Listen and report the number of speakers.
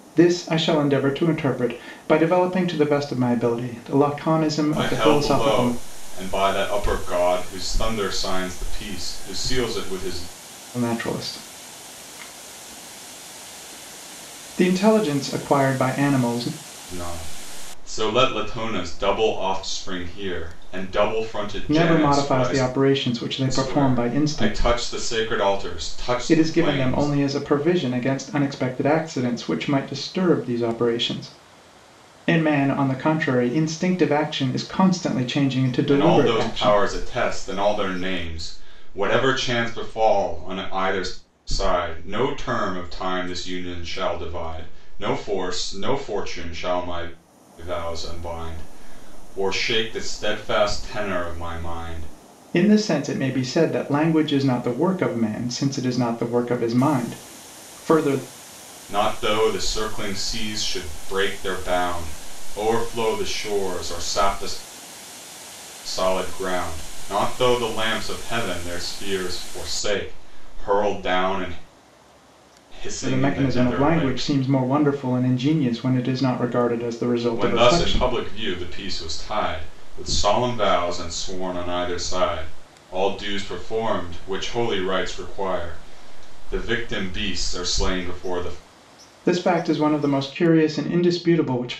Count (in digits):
2